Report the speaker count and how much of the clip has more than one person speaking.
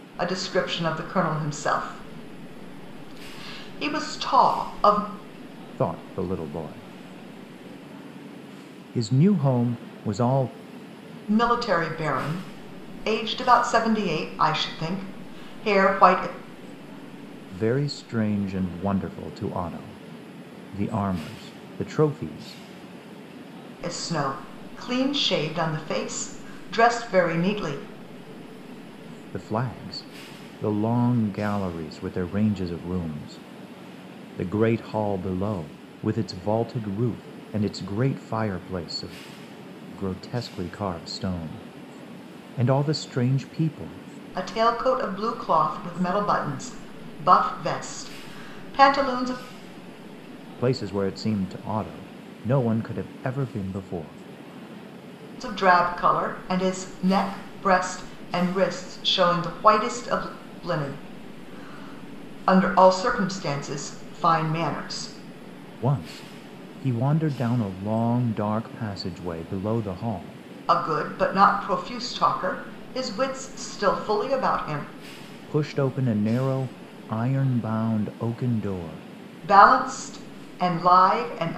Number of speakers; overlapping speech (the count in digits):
2, no overlap